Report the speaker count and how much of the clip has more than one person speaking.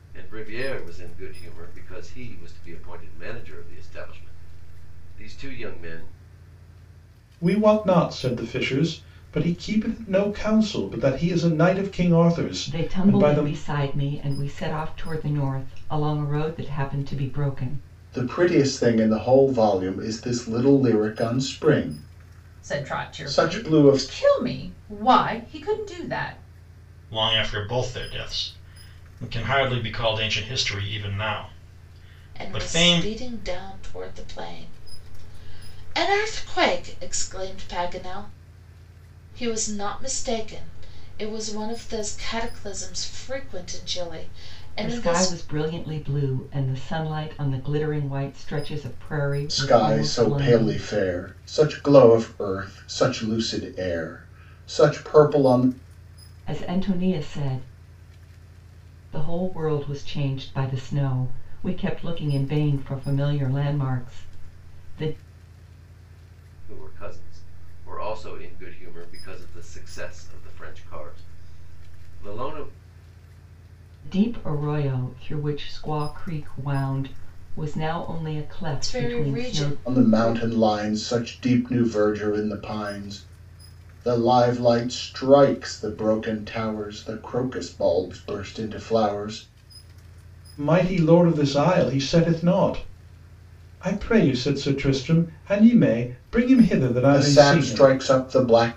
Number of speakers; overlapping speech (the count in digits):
7, about 8%